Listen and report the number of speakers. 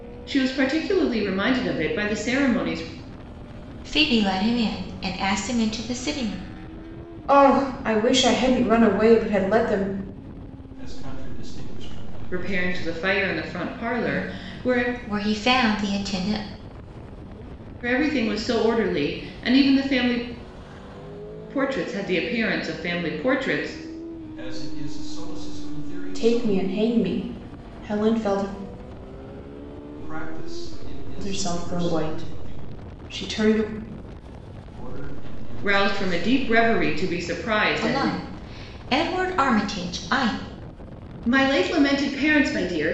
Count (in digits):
4